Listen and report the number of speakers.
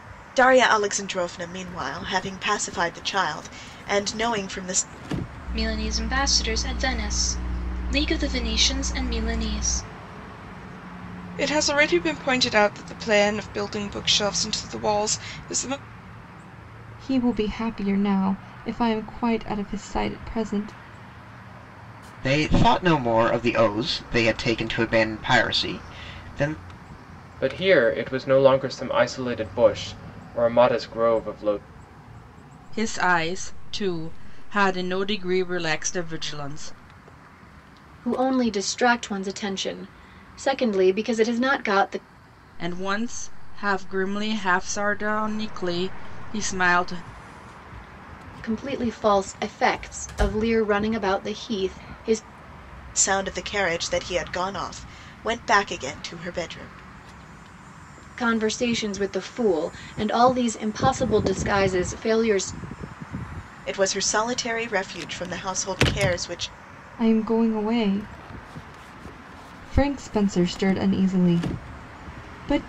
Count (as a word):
eight